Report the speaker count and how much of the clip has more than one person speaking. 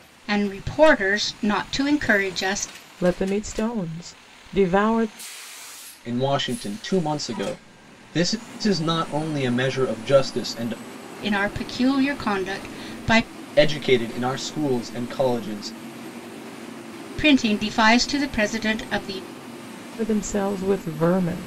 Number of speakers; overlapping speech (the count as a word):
three, no overlap